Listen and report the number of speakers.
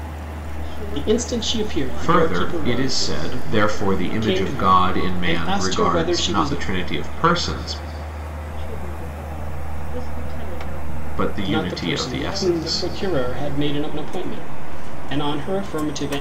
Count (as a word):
three